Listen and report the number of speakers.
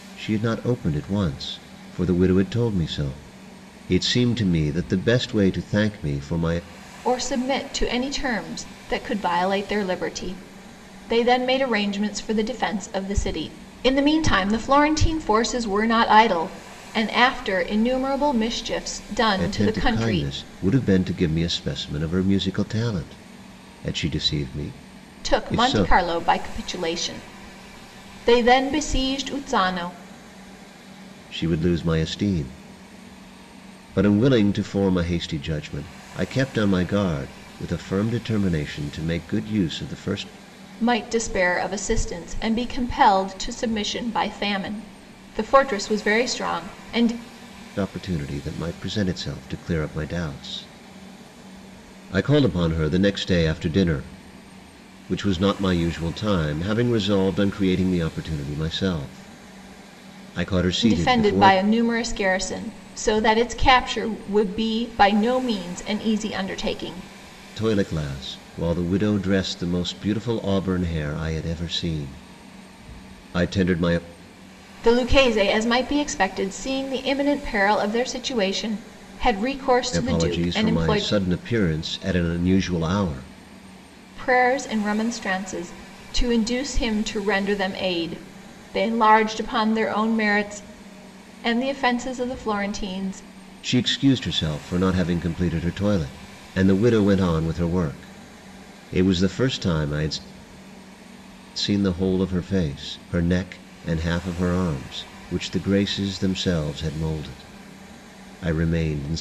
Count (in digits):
2